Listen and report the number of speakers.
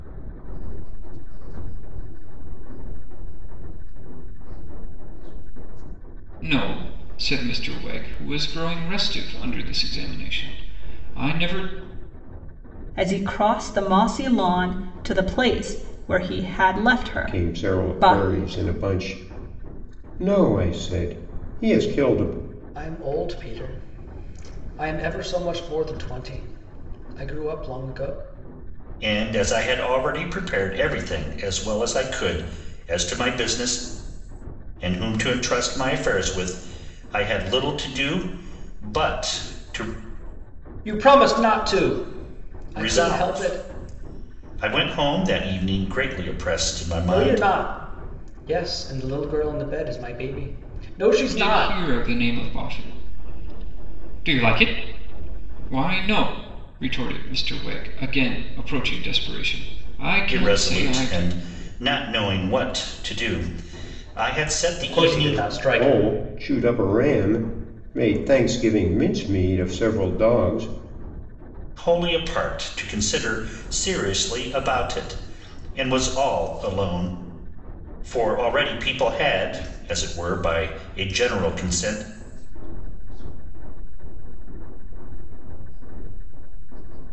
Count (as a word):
six